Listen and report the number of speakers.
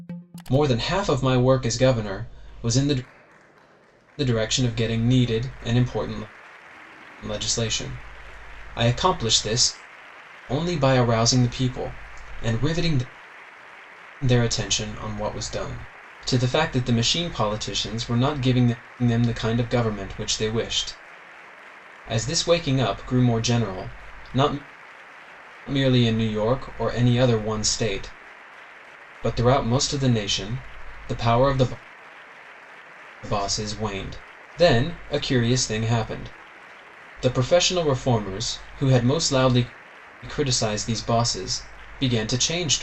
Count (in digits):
1